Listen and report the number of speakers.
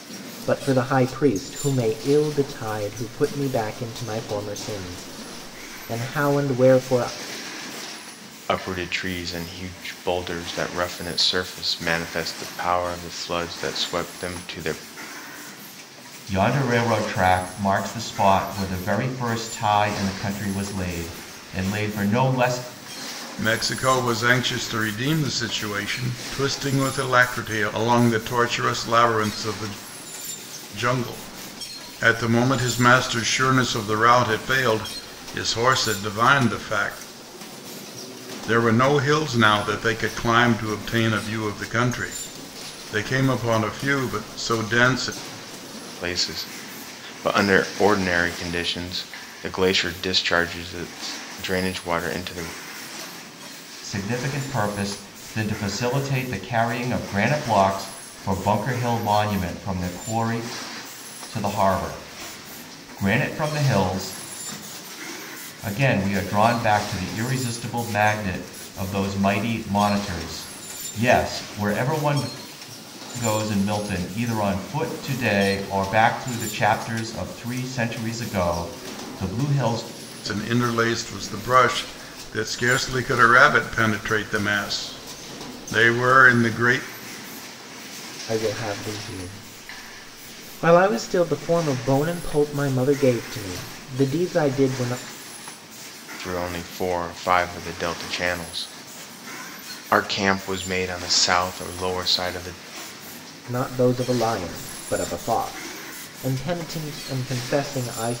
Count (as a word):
four